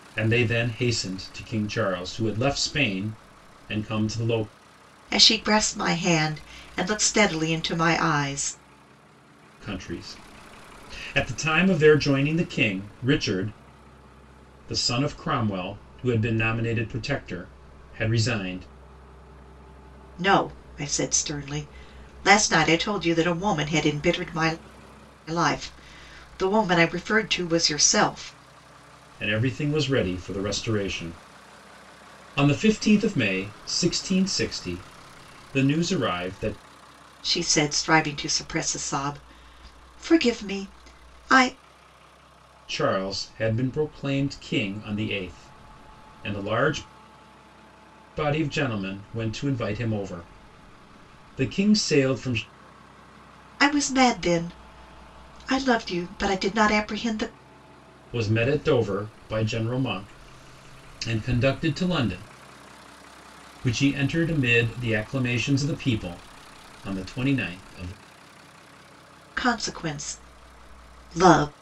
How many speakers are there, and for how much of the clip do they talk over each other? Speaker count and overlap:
two, no overlap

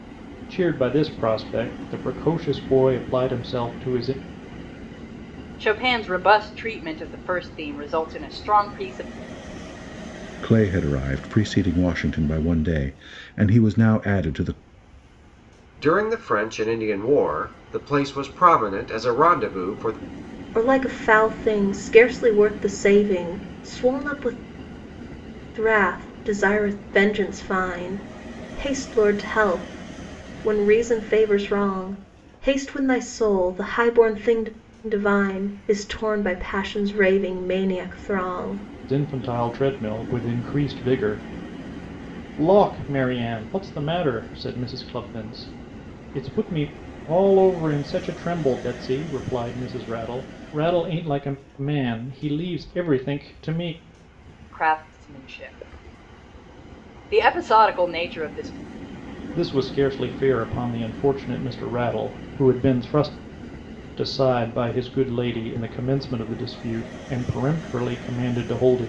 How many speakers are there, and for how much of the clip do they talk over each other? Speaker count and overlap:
five, no overlap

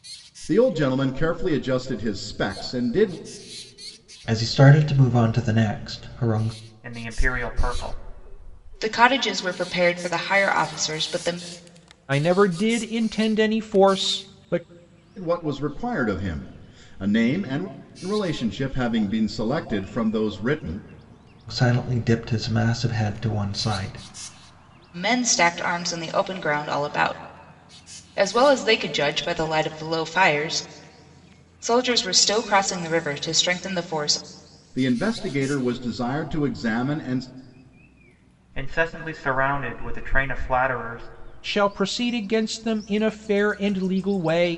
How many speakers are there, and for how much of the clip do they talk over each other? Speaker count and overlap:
five, no overlap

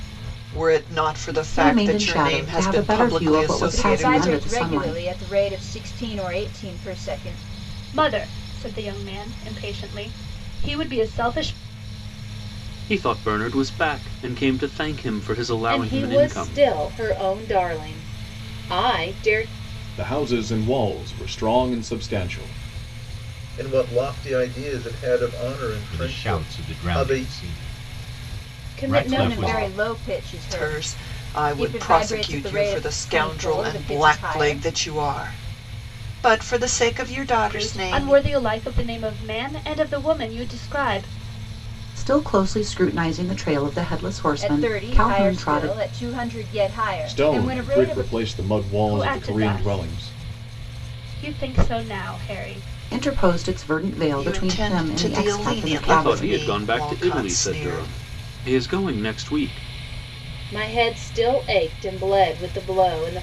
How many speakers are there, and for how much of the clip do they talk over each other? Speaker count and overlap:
nine, about 31%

